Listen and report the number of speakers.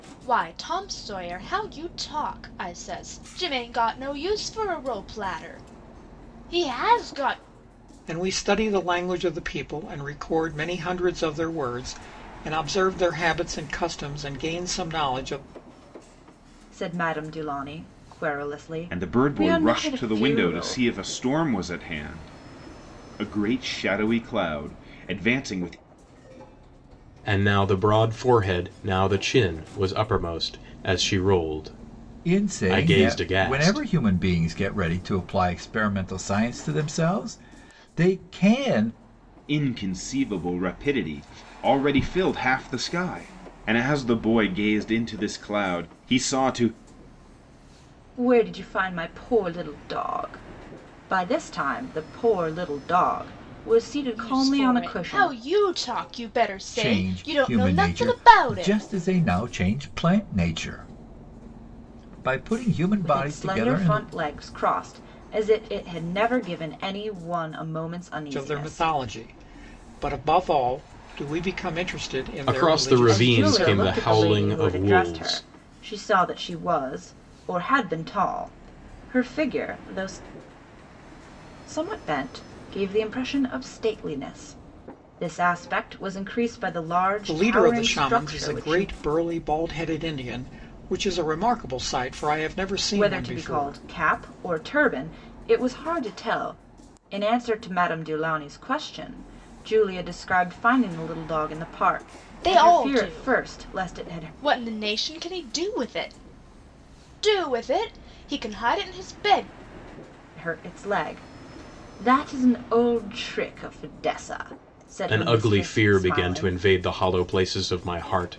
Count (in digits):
6